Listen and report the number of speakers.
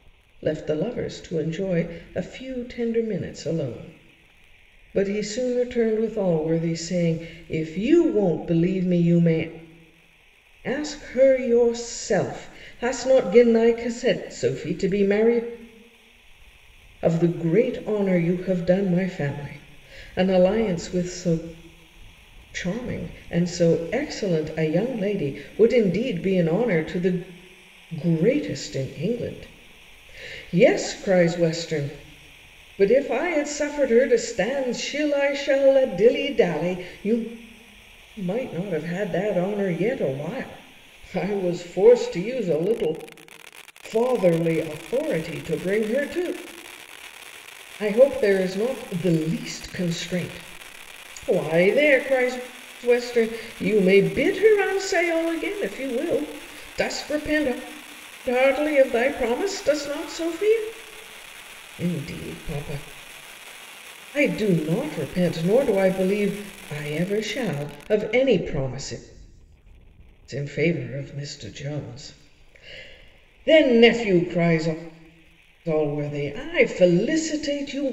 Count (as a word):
one